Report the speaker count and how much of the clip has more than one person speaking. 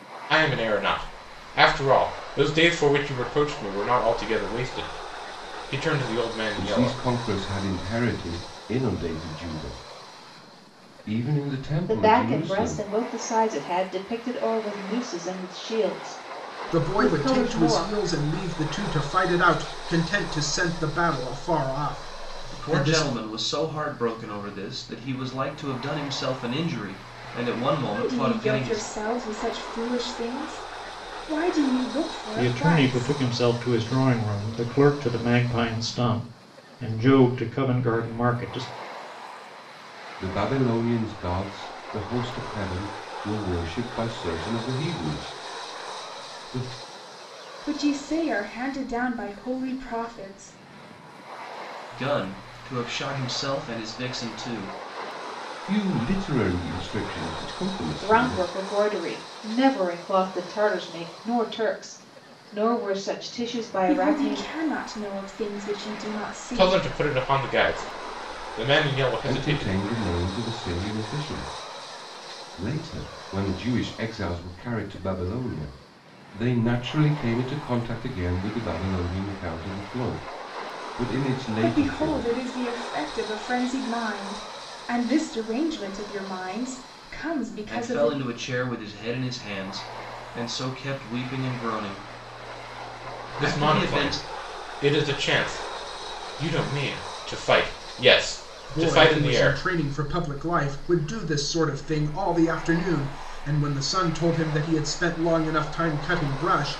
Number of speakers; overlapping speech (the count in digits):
7, about 10%